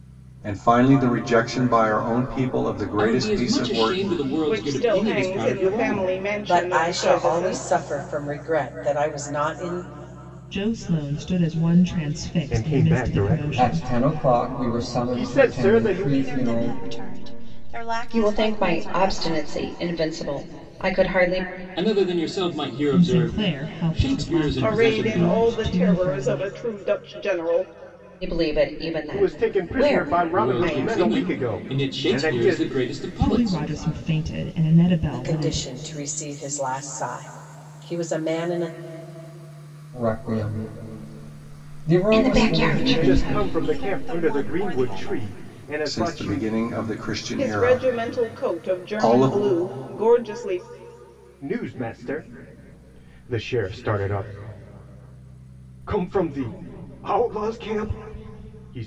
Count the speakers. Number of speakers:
9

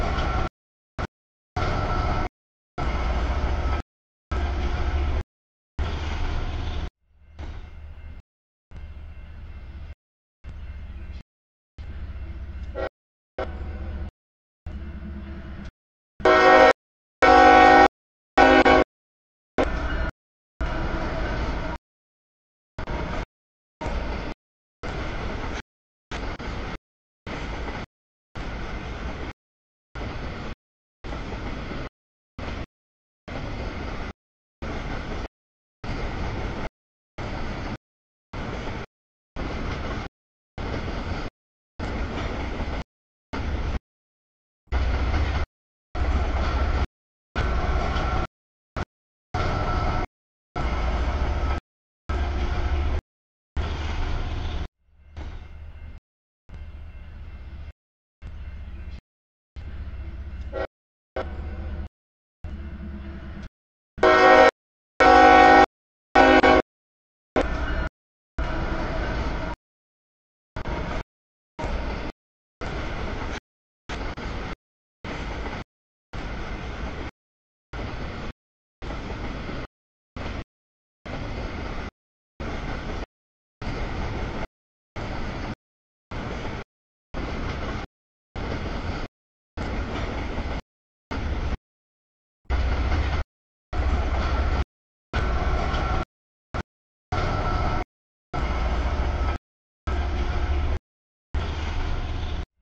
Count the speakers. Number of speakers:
0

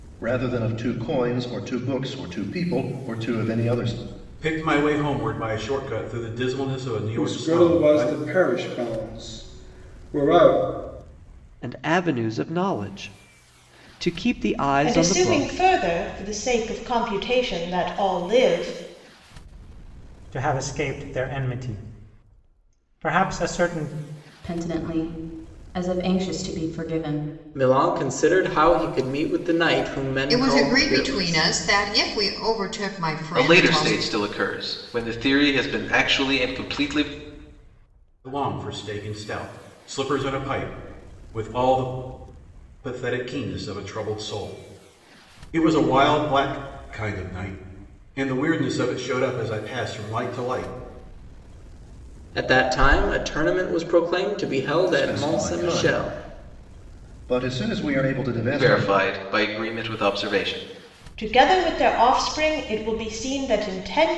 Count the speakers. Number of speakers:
10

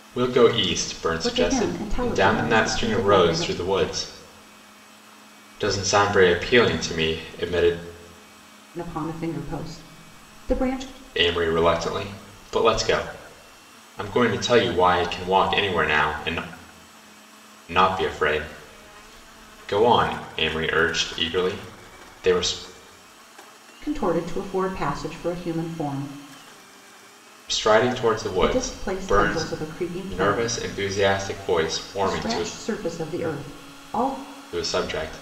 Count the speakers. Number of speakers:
2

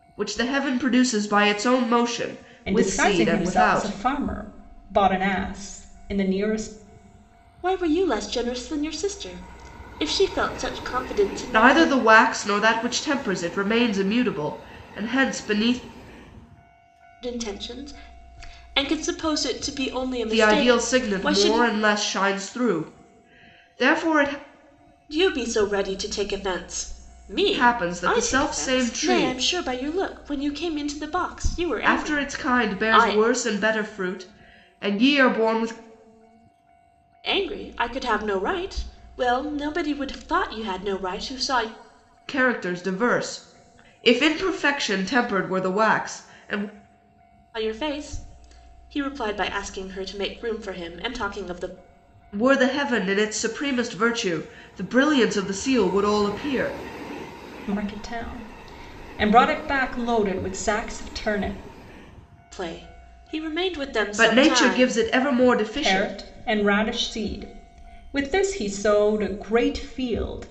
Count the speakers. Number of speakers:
3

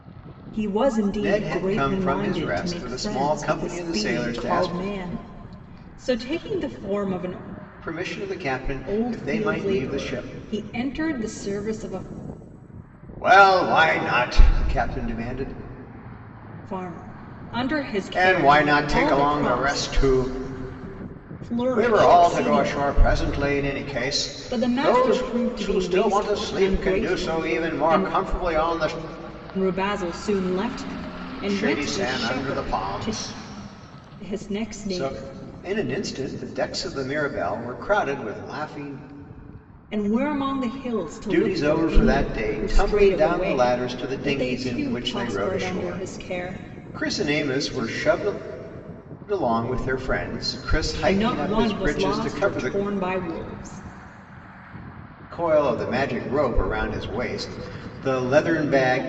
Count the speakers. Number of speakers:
2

